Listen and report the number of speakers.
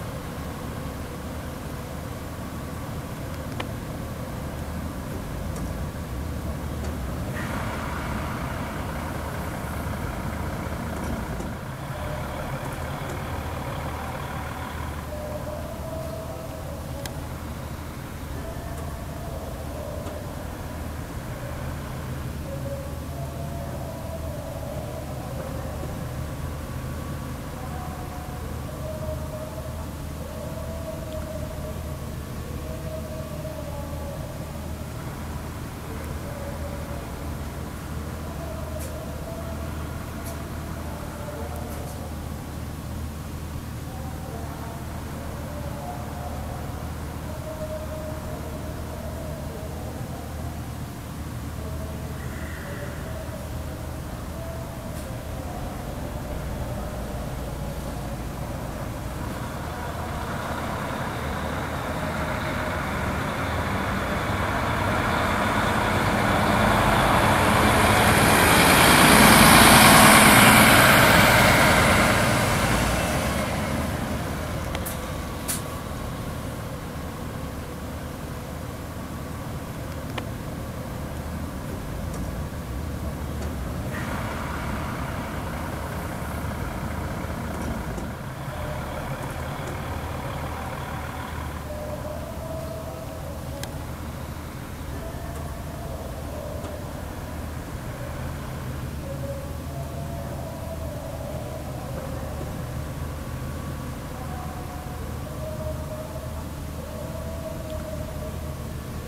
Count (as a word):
zero